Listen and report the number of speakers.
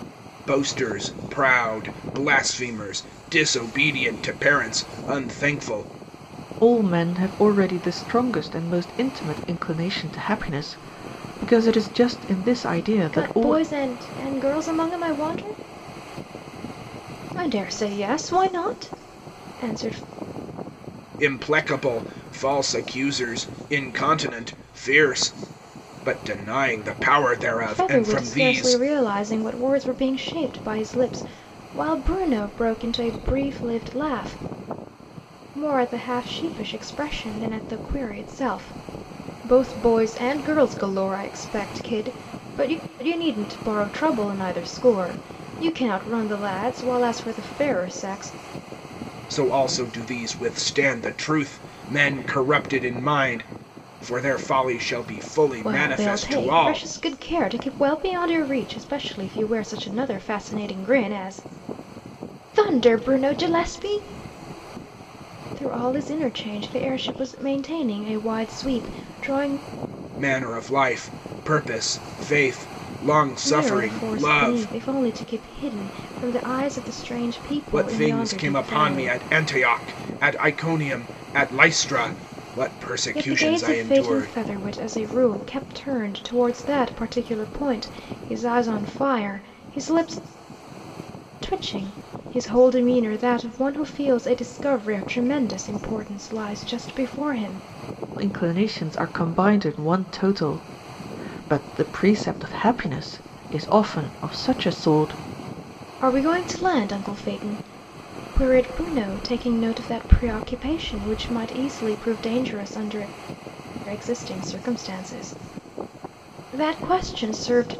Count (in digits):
3